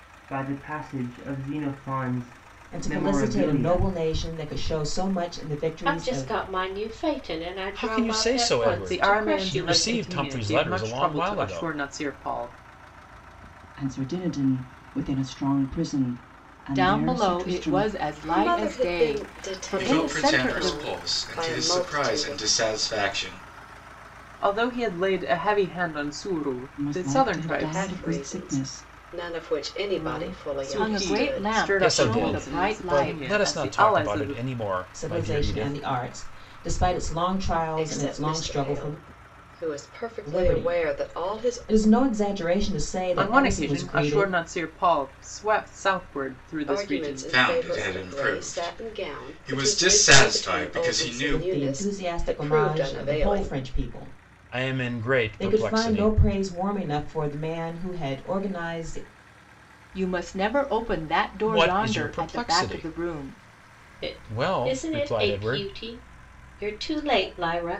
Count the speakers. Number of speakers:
nine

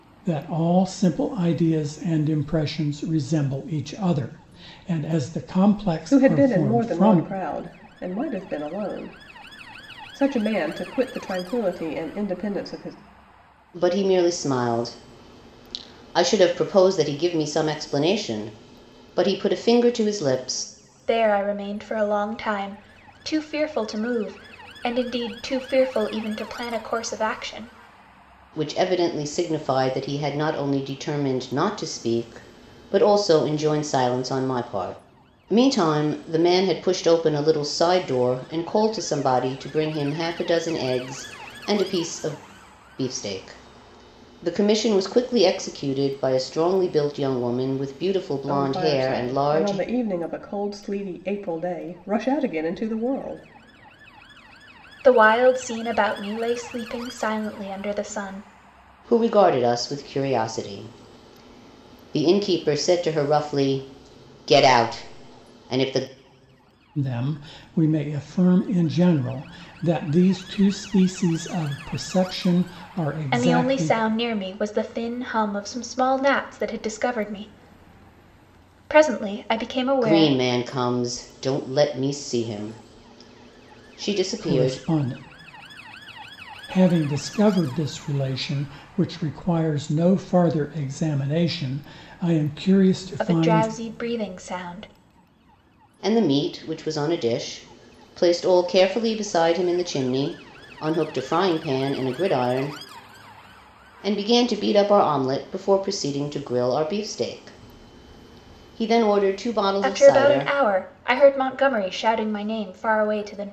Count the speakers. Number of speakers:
four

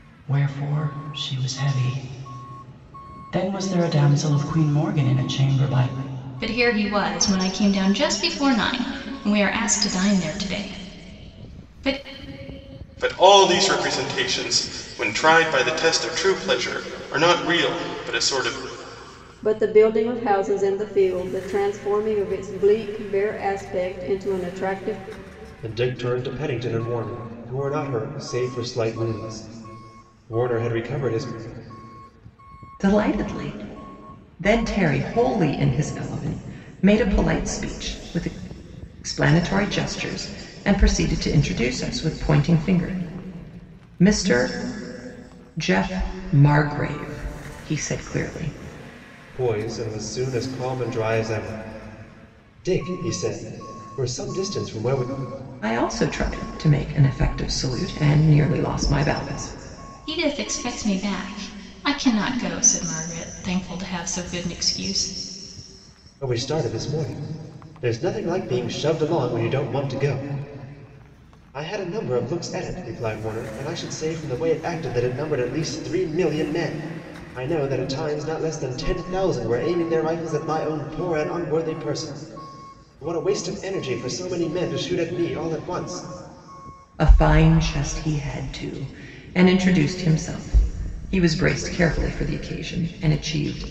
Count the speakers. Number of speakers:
six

